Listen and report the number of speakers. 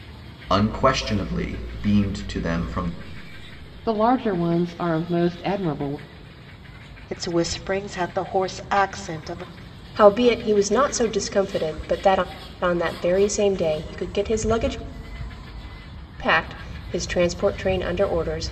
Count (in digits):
4